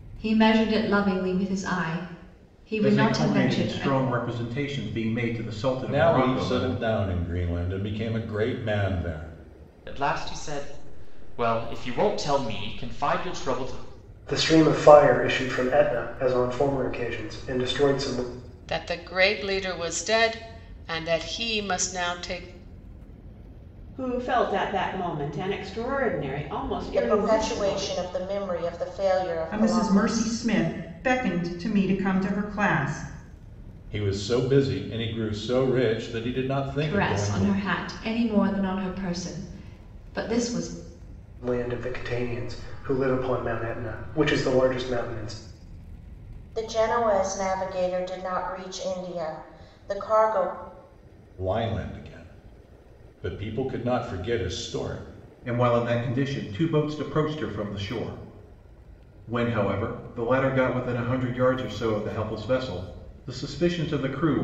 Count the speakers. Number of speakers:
9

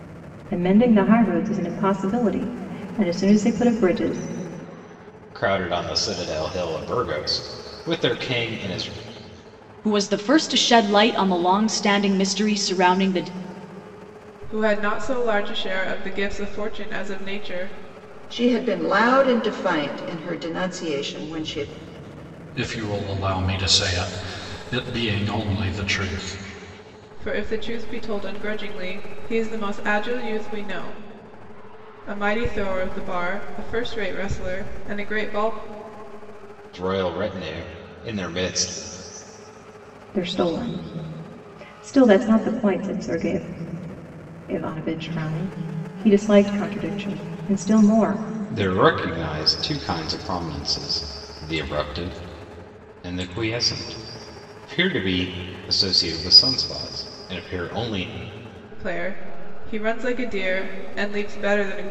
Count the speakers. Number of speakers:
6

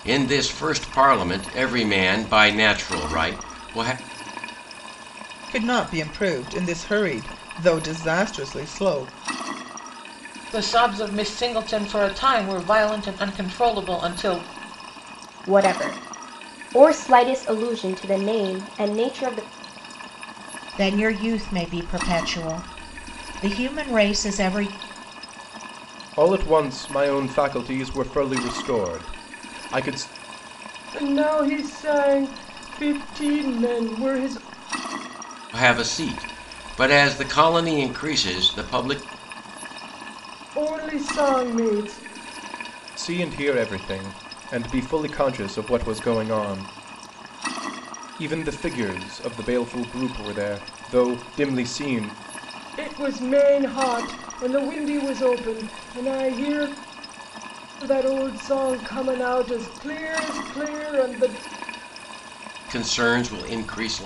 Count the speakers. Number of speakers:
7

